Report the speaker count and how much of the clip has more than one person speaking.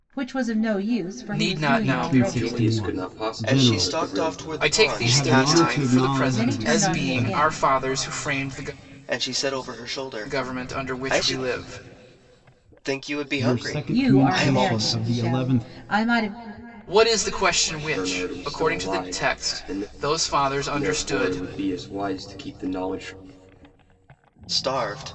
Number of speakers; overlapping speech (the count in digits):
5, about 49%